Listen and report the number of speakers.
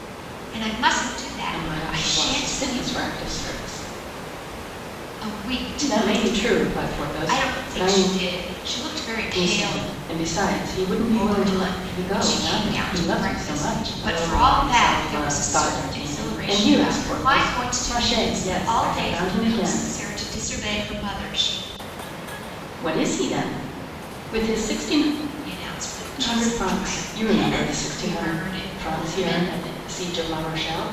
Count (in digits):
2